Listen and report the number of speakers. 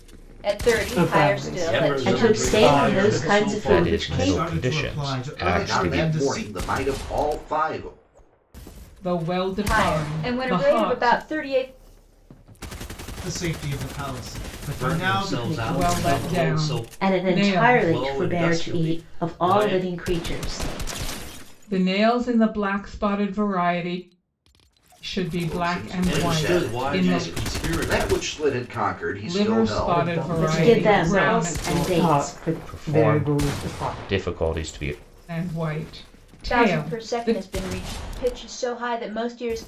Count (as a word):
eight